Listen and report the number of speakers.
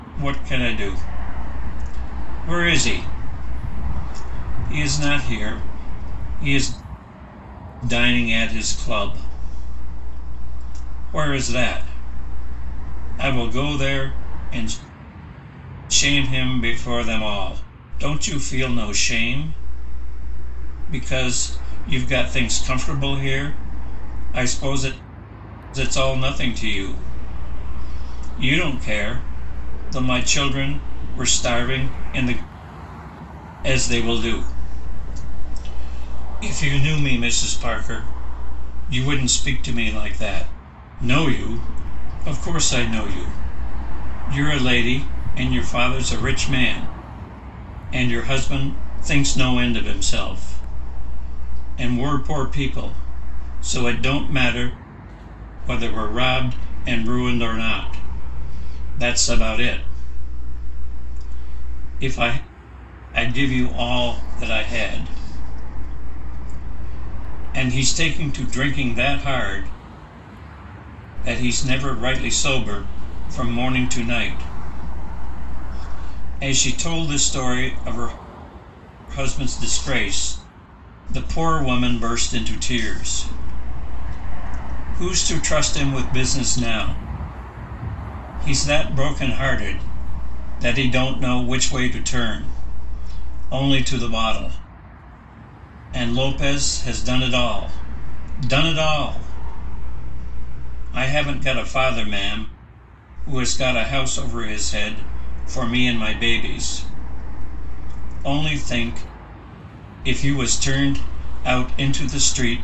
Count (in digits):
1